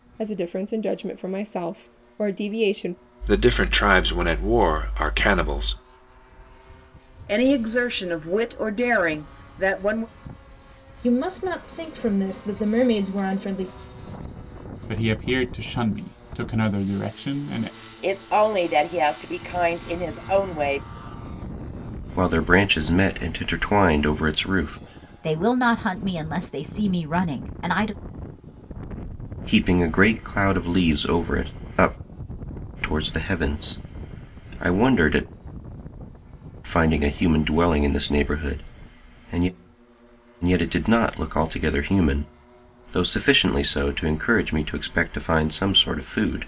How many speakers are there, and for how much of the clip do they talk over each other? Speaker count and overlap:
8, no overlap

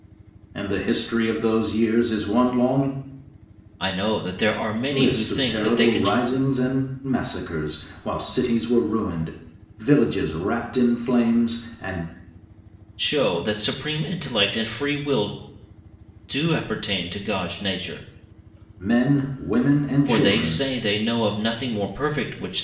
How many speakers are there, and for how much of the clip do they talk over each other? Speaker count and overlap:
2, about 8%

